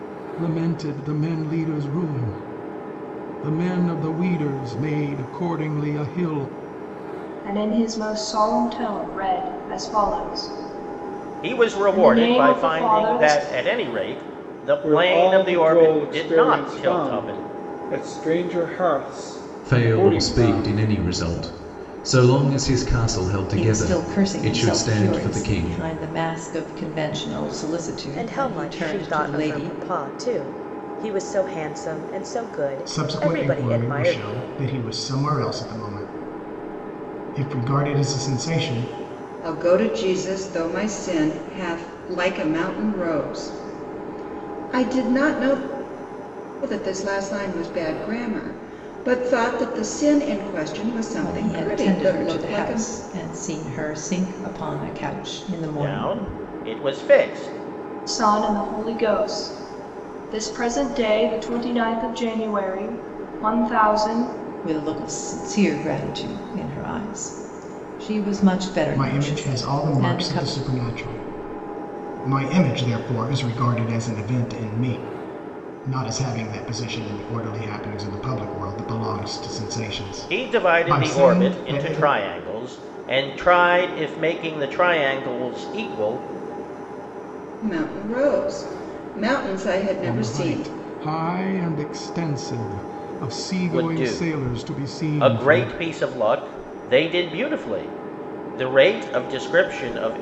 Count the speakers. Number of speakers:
9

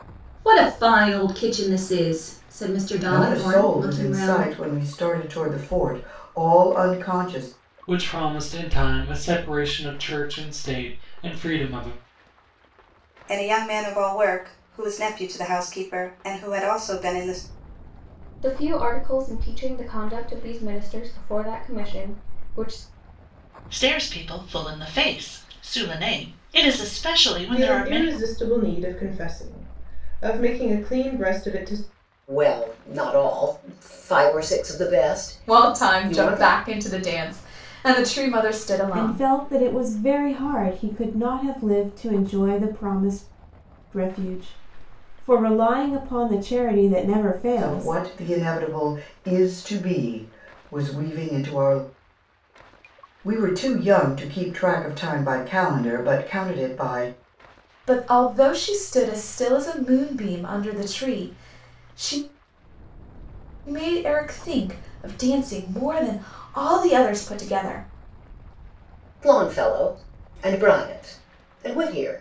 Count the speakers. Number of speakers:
10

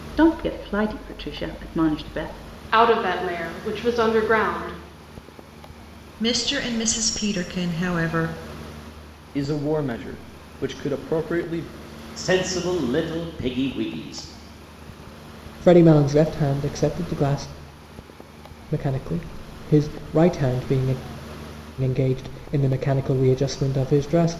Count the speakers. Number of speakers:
6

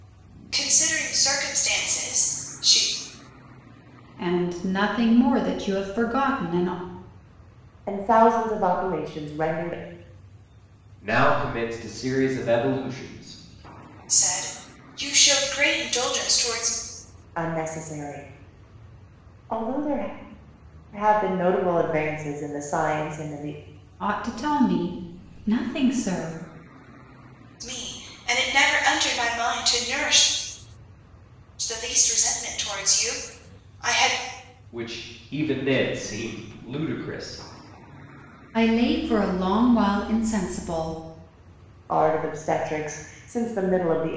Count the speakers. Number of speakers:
4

